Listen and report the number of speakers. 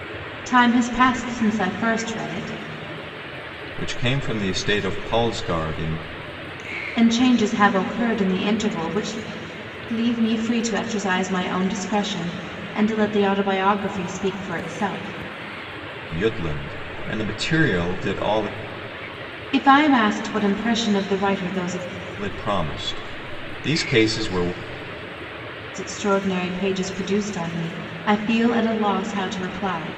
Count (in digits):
2